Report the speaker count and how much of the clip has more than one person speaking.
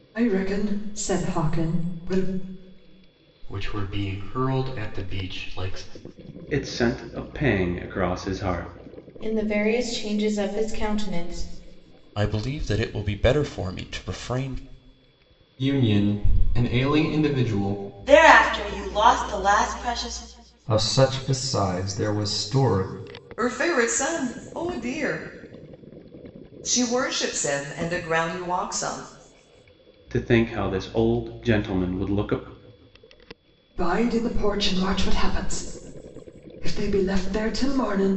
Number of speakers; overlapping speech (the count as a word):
nine, no overlap